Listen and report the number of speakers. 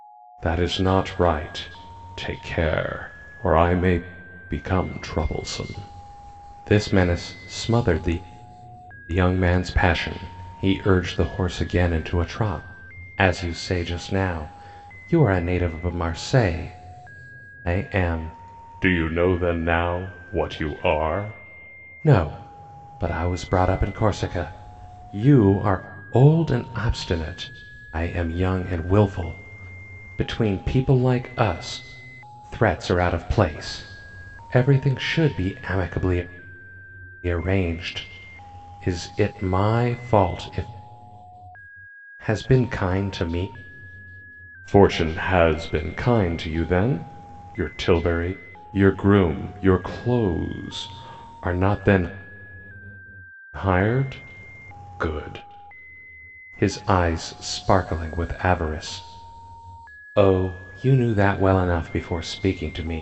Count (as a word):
one